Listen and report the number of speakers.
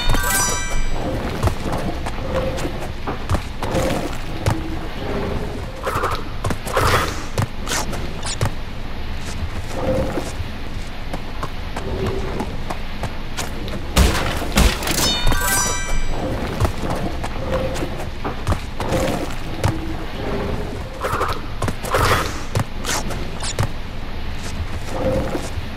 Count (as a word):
zero